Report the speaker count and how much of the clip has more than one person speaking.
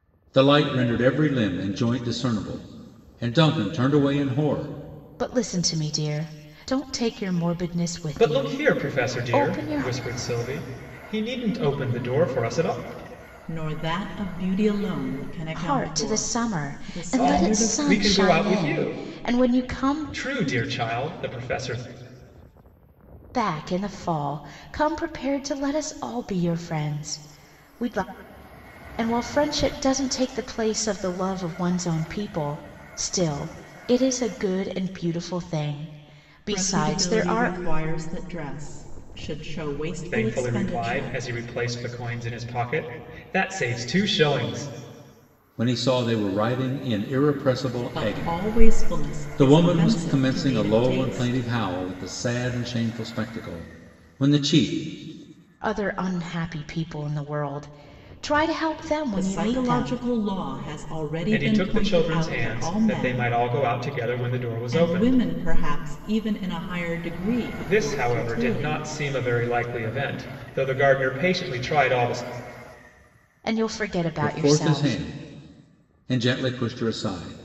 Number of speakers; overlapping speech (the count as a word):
four, about 23%